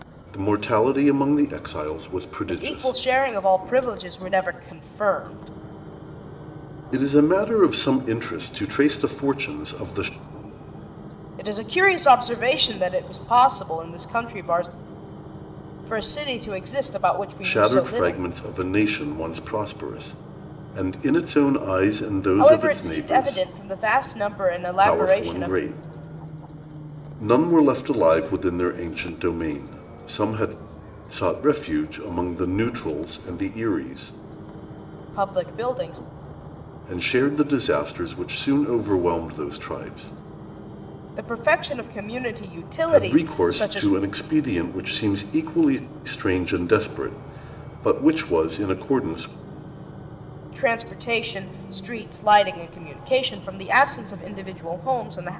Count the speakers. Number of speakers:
2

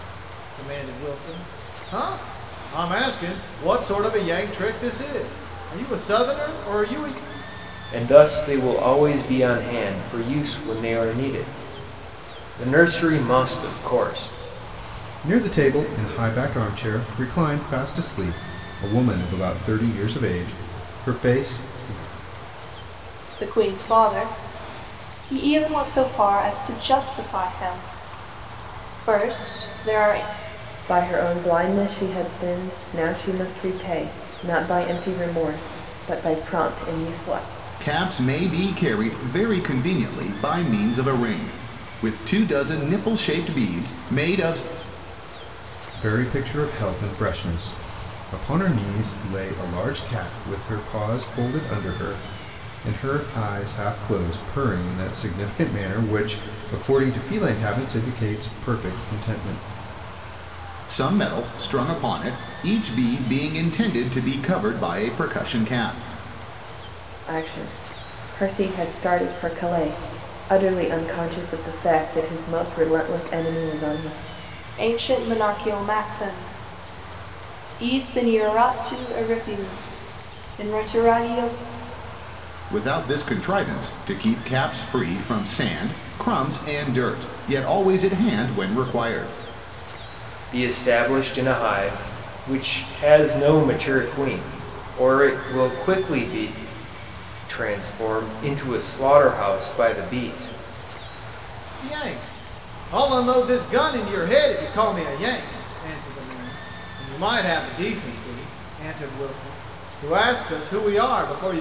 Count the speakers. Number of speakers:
6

